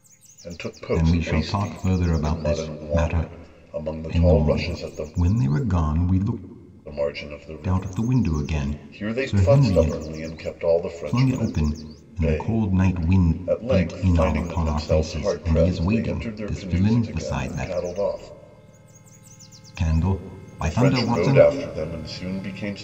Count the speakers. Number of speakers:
2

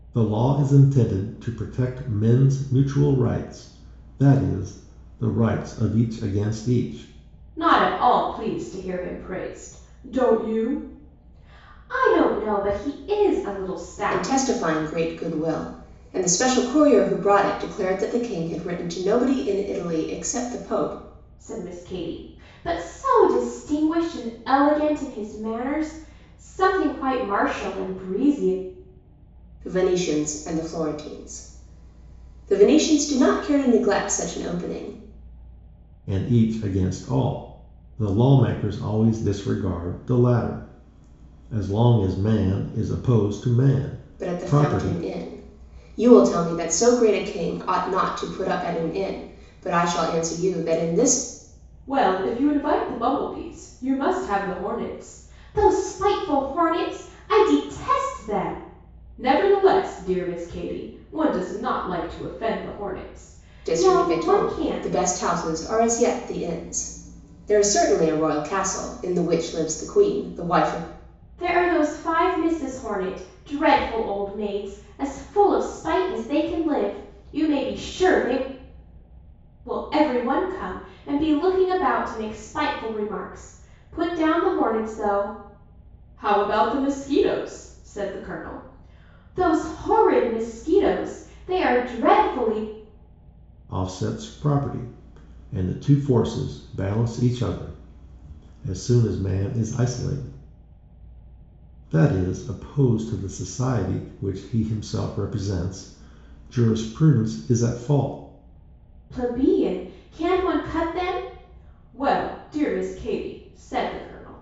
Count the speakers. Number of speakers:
3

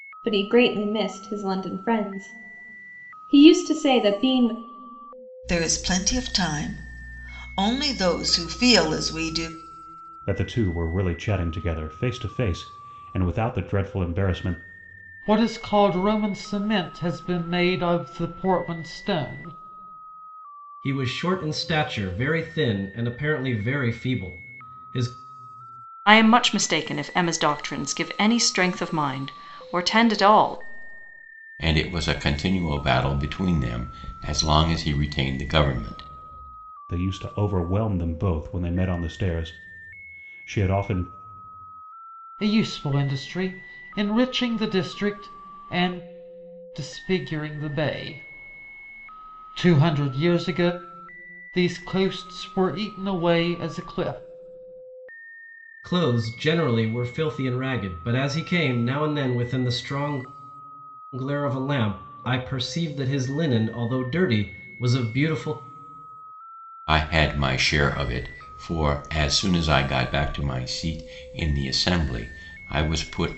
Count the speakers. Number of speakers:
7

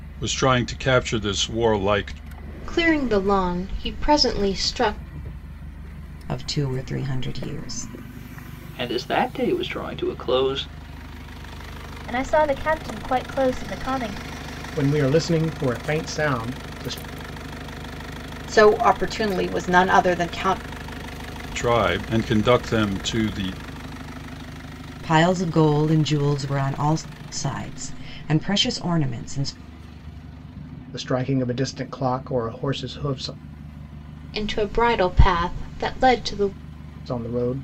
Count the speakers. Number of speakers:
7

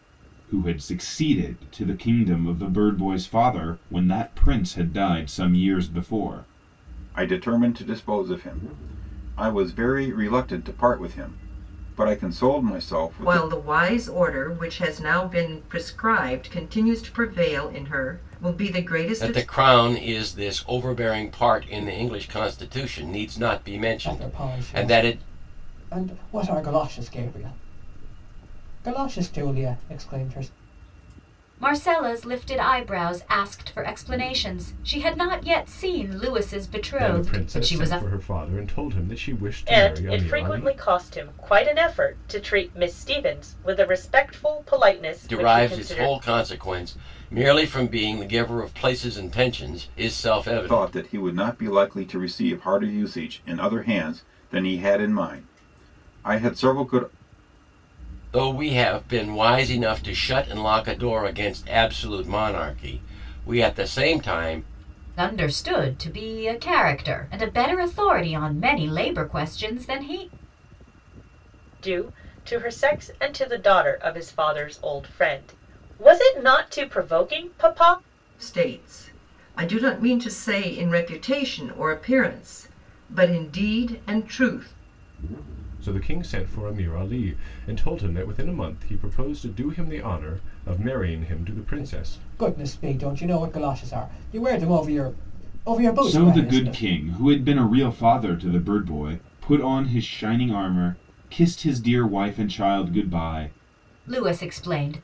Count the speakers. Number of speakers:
8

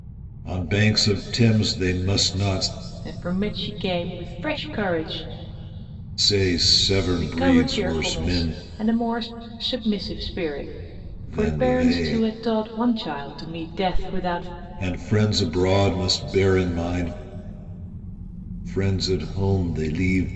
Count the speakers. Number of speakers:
2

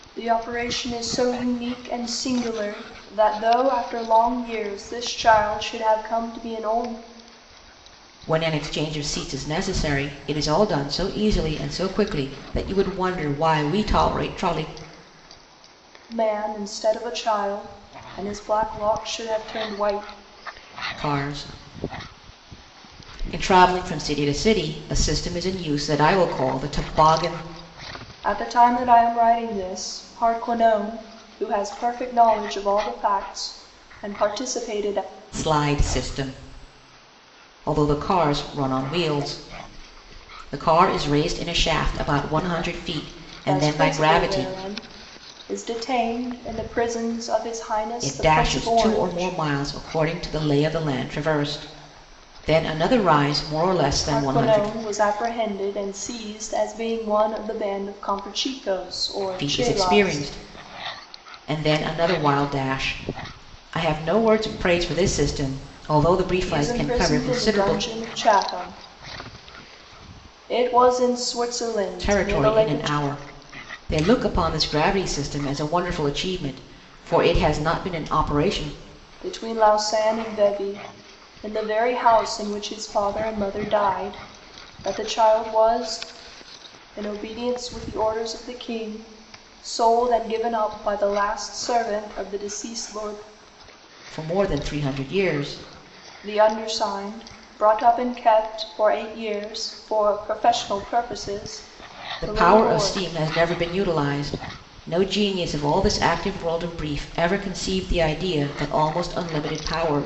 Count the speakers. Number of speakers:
2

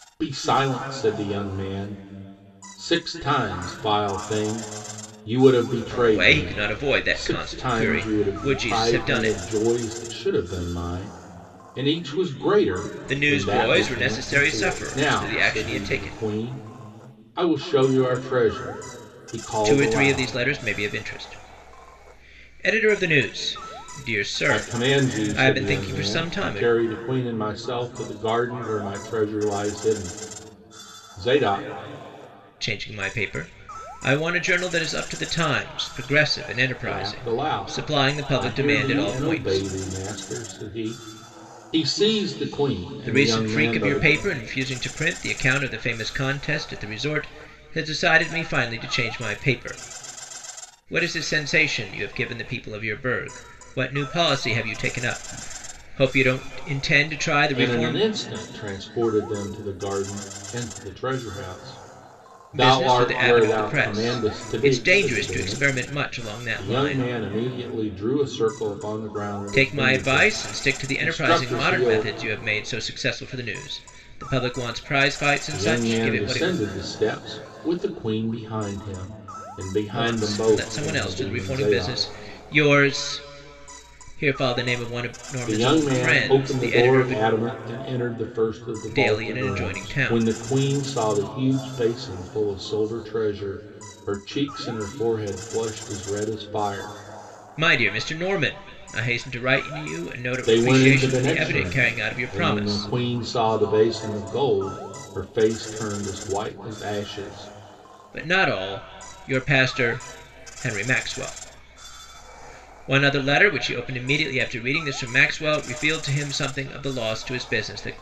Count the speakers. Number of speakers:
2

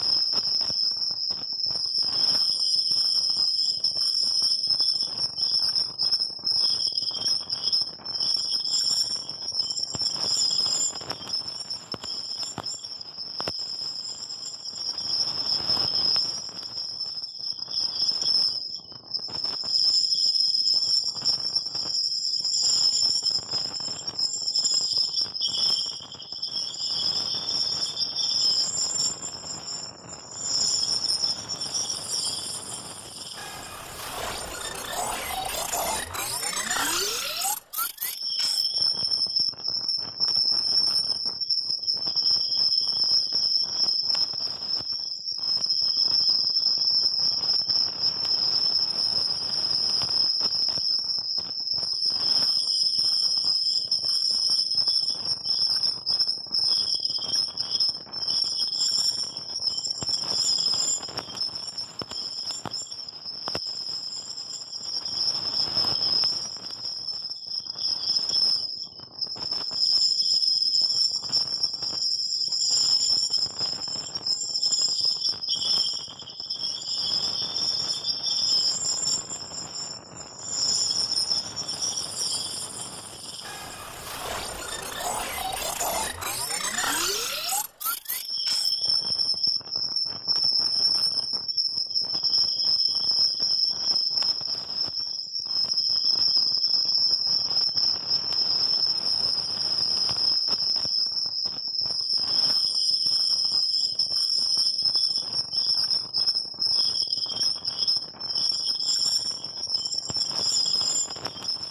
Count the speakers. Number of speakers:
0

